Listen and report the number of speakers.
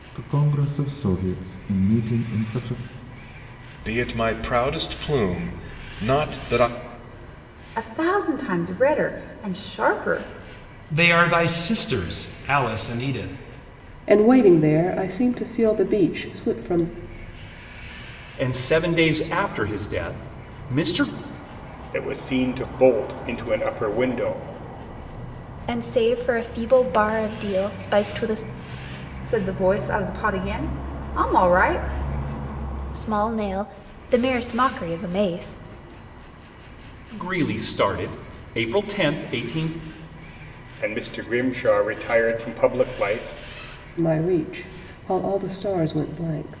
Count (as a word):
eight